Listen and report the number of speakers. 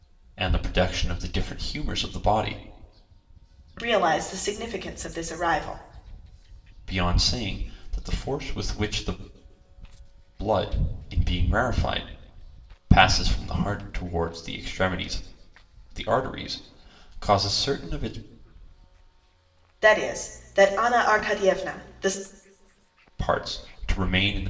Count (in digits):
2